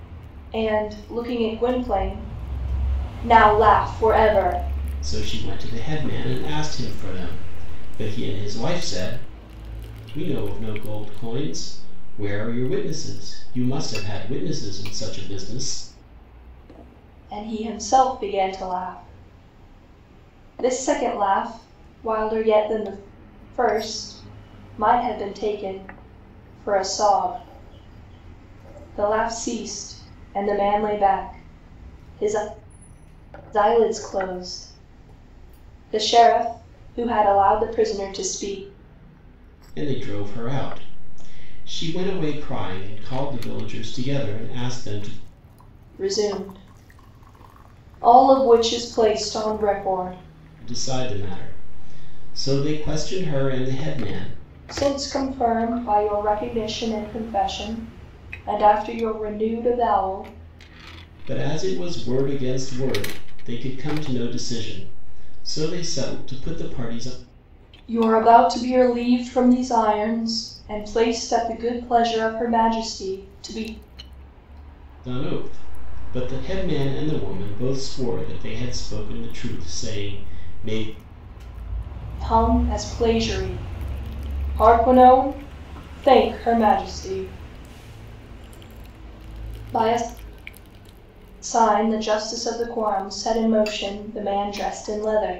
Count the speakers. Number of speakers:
2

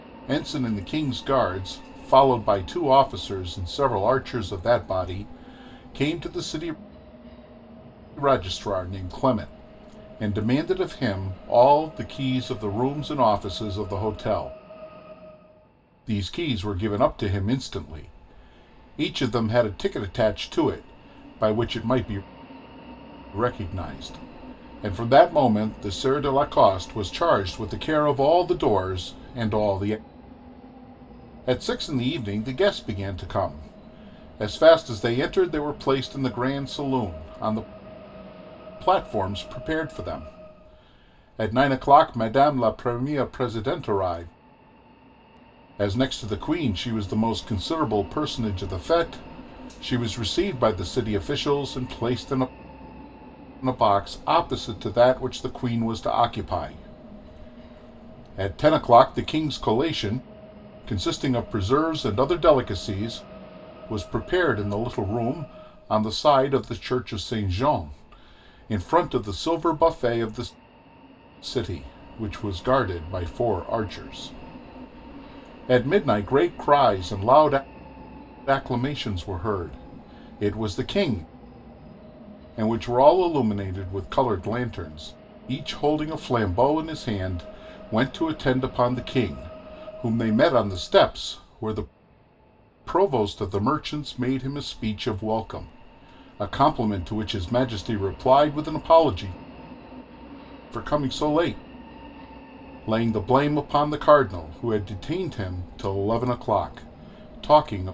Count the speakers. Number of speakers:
1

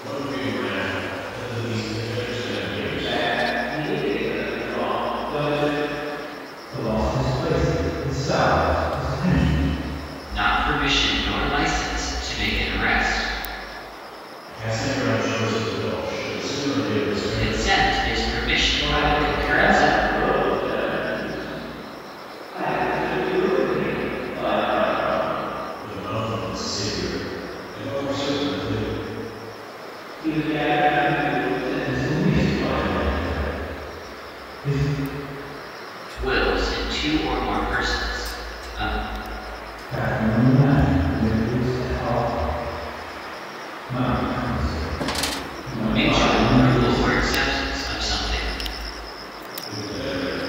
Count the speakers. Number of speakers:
4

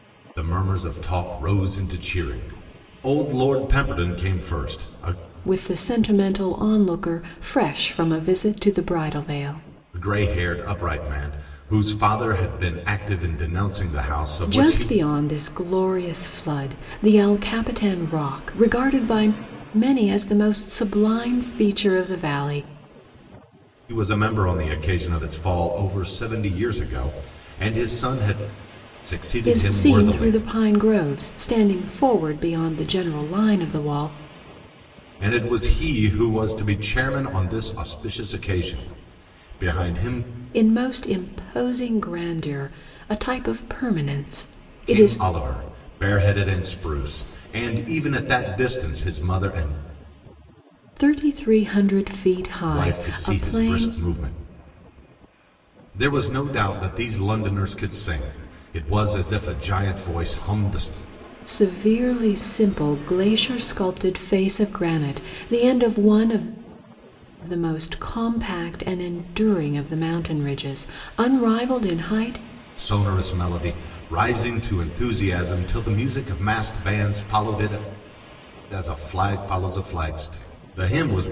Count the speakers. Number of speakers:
2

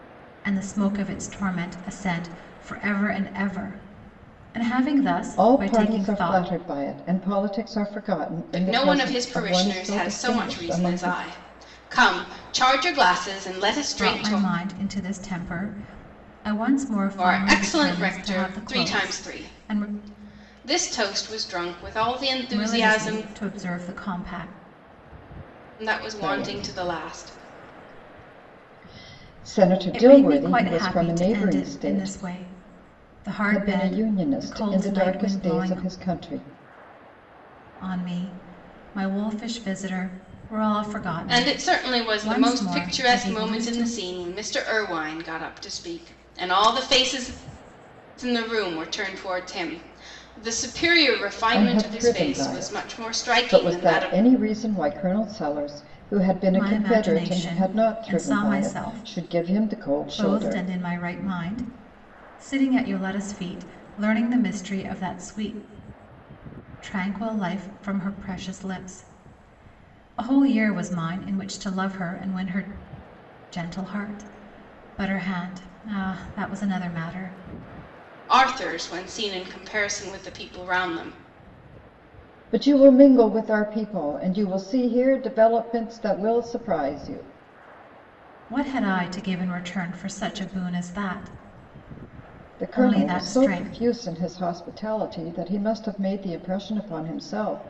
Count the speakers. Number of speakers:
3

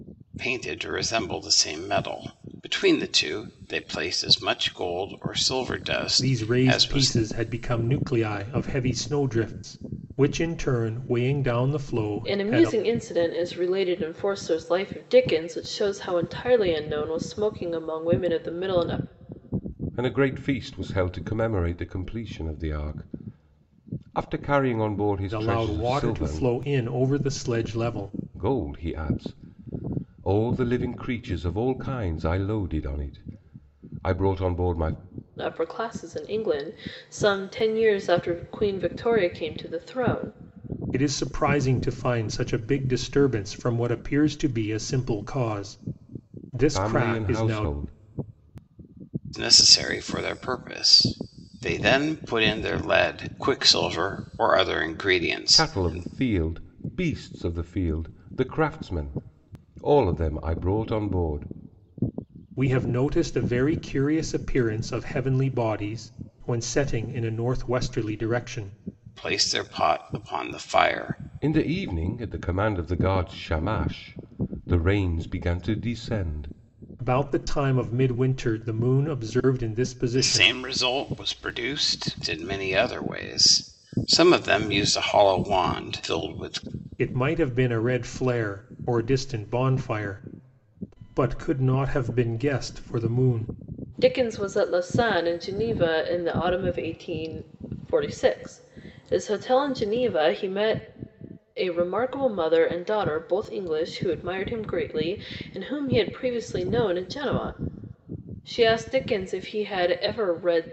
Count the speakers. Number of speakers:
4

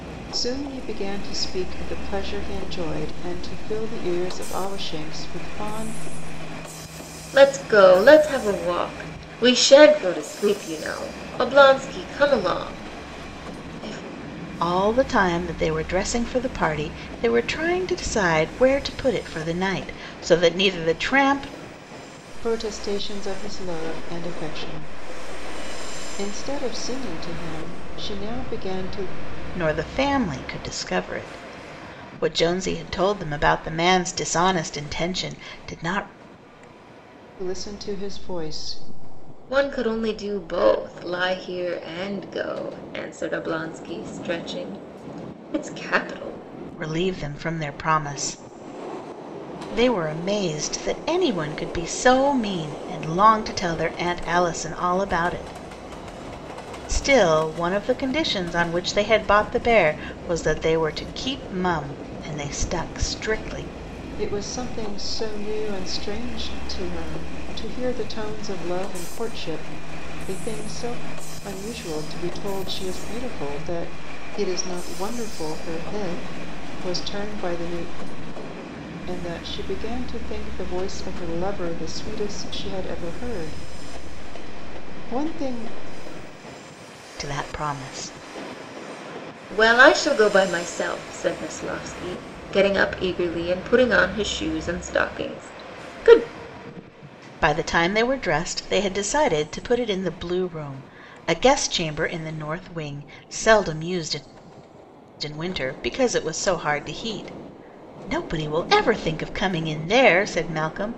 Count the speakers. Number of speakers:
3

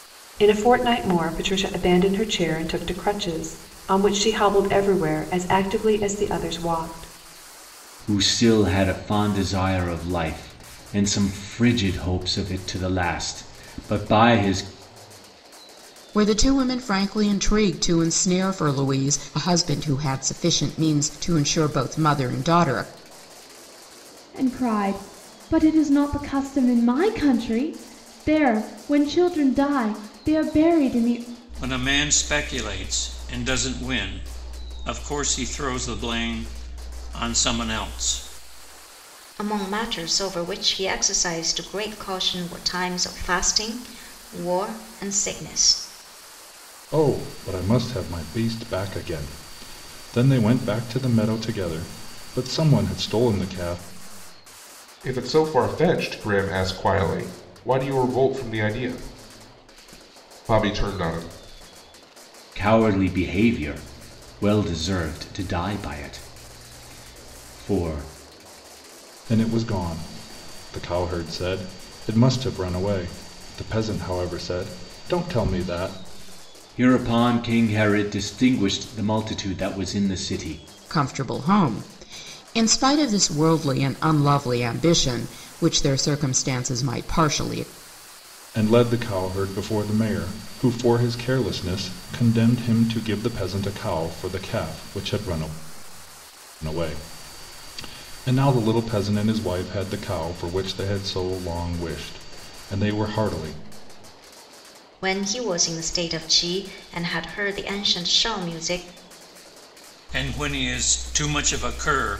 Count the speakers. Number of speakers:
8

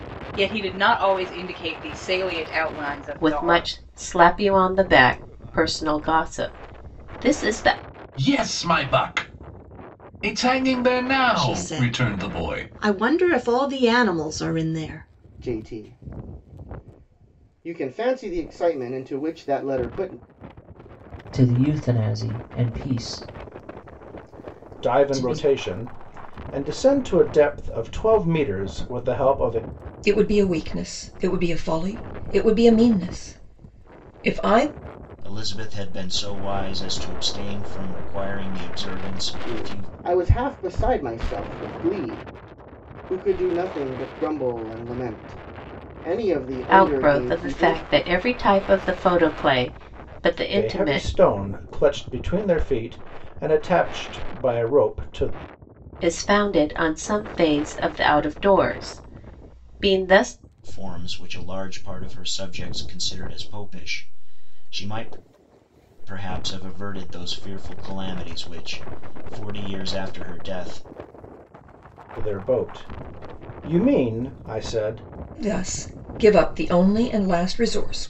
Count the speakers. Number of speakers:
9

